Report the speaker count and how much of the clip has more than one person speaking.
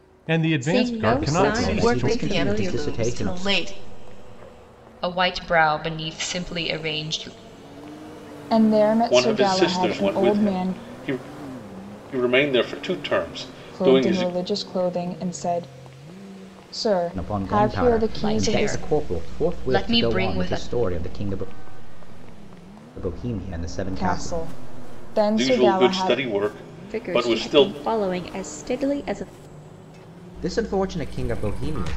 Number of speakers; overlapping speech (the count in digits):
7, about 34%